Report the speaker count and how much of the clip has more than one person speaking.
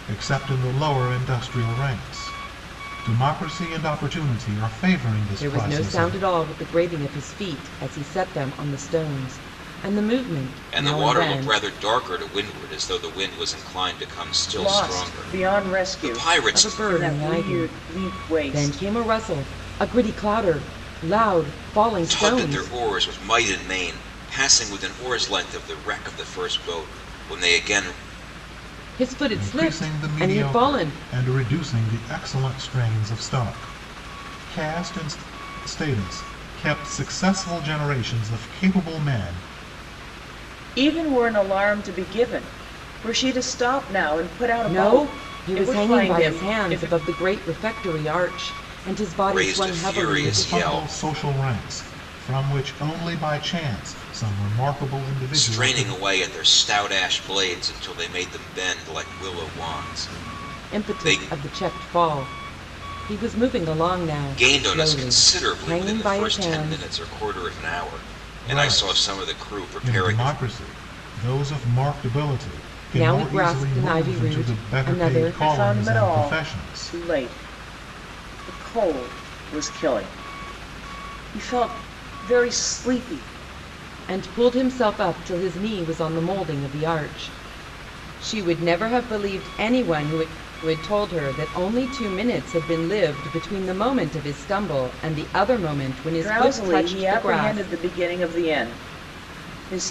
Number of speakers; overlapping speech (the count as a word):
four, about 23%